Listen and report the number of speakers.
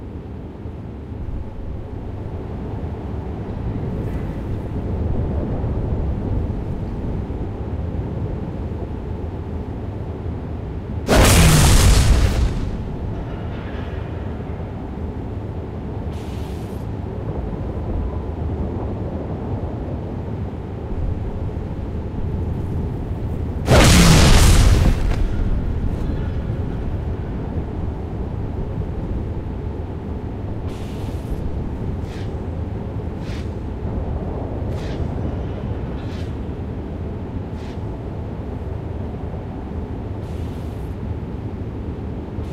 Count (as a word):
zero